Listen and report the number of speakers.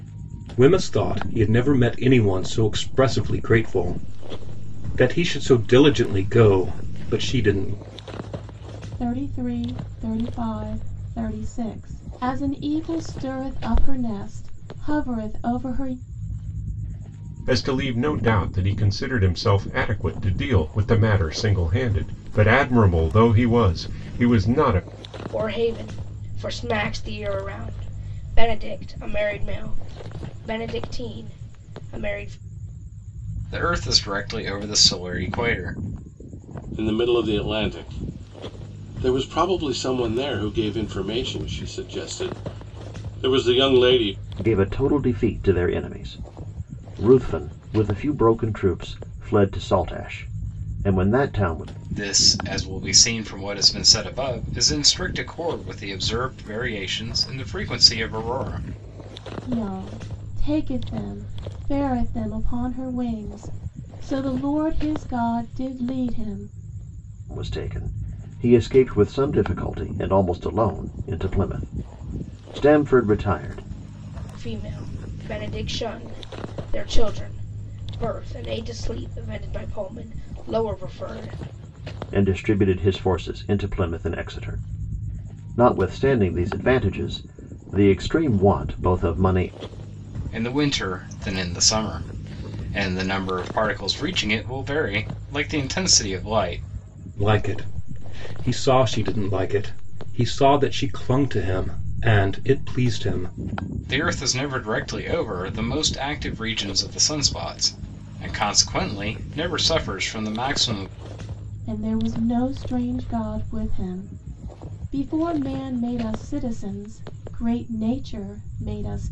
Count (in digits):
7